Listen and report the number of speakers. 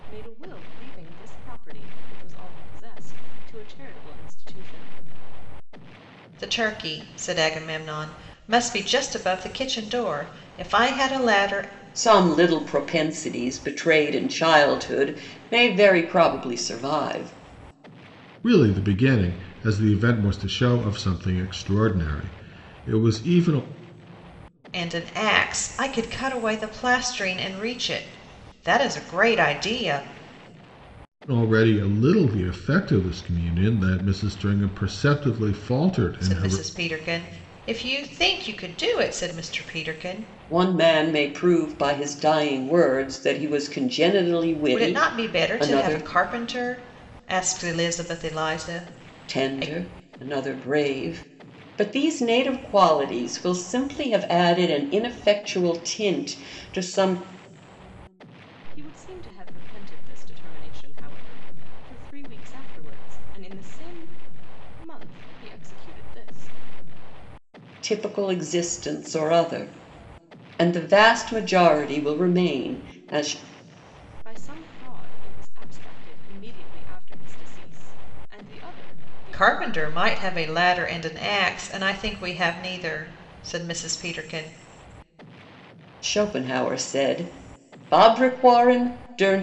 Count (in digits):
4